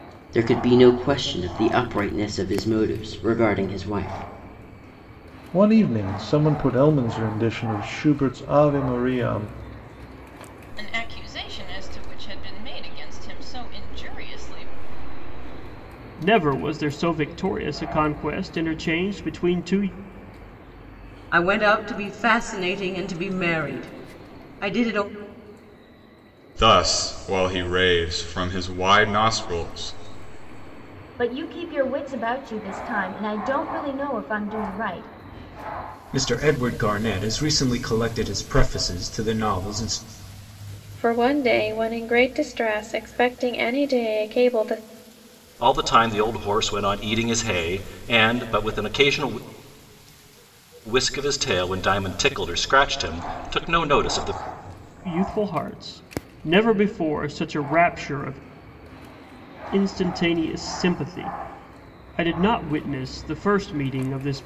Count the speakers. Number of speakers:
10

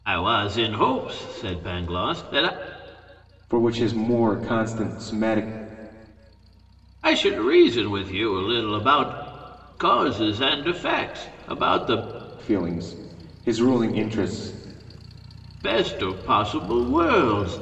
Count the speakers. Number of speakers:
2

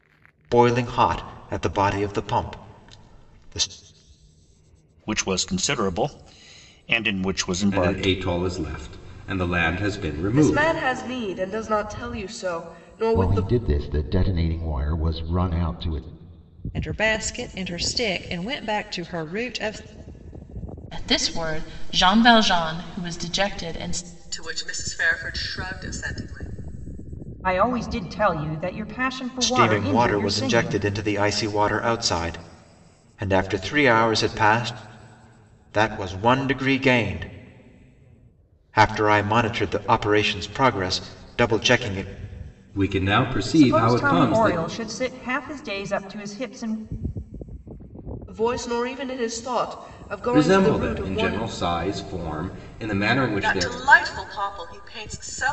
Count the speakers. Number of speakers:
9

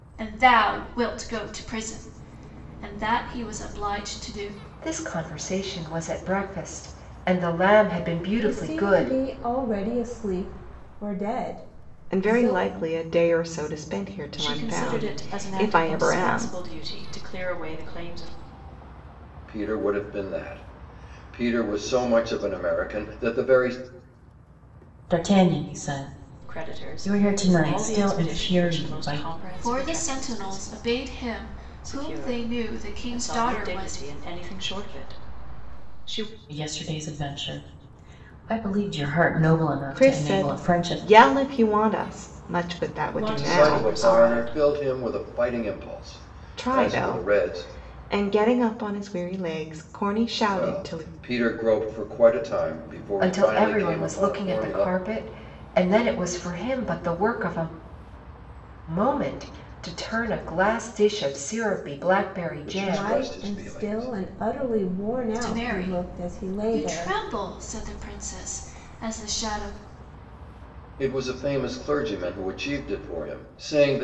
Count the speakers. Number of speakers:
7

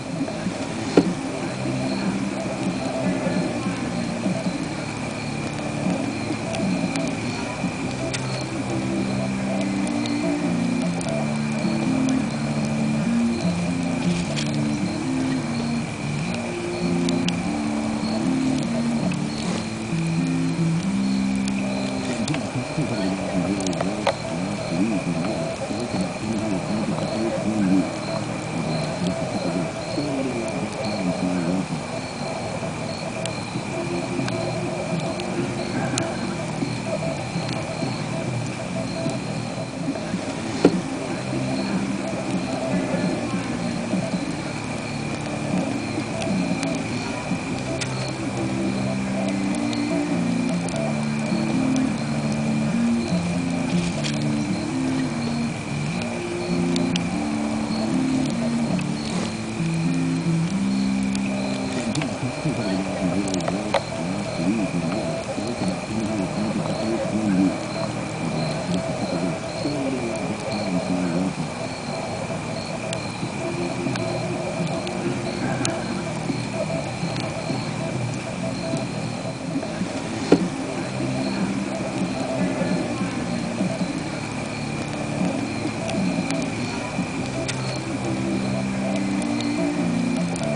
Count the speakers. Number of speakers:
0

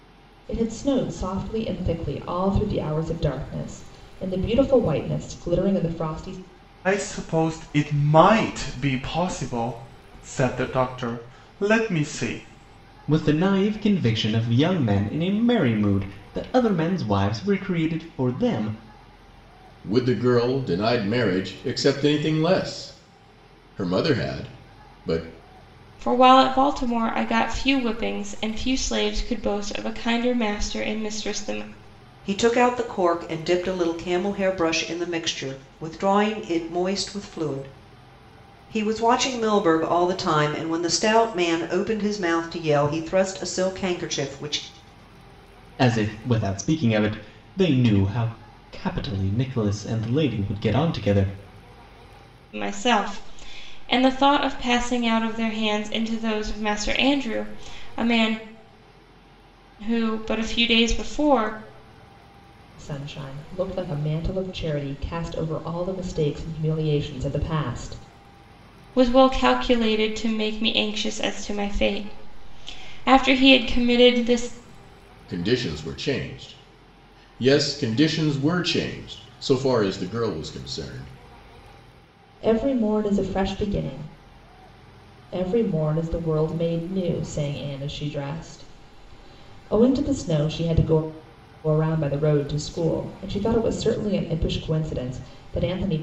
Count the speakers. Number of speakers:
6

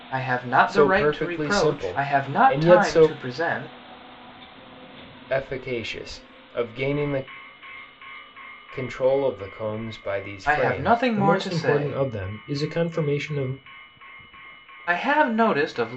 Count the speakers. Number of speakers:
2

